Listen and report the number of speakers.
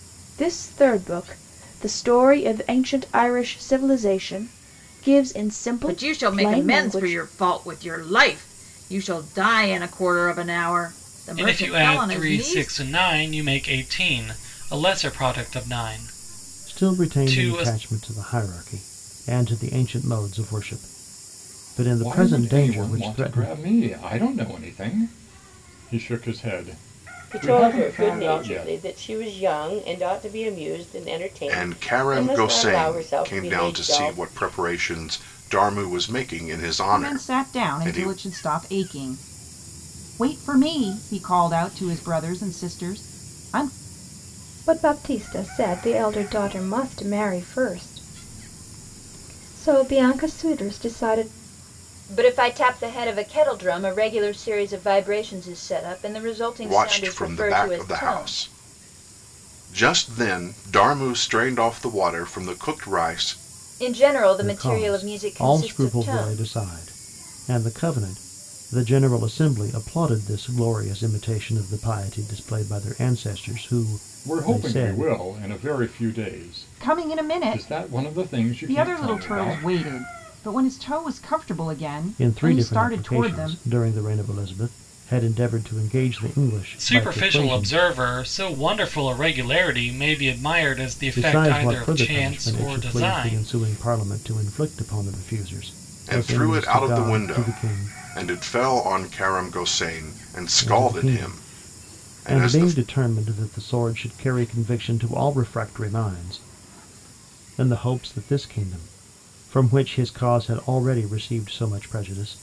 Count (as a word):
ten